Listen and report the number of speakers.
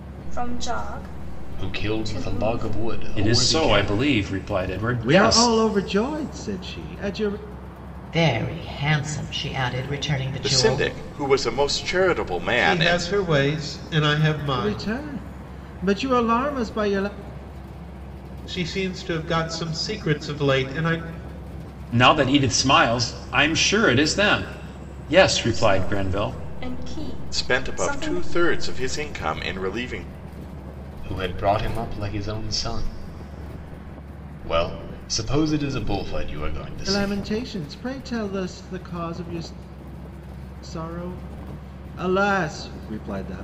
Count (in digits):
7